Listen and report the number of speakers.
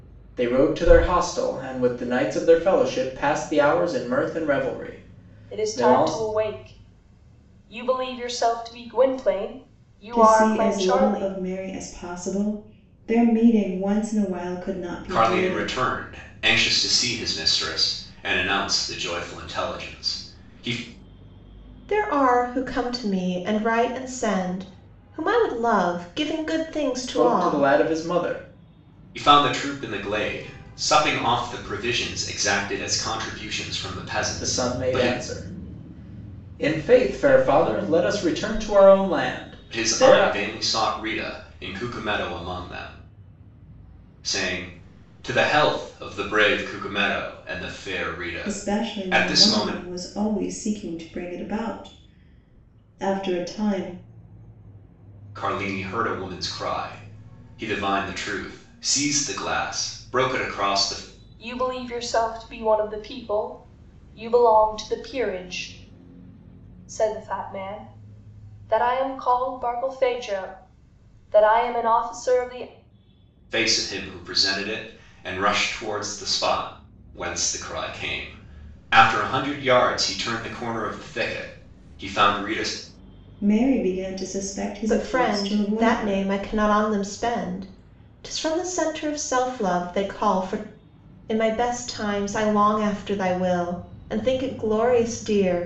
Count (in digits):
5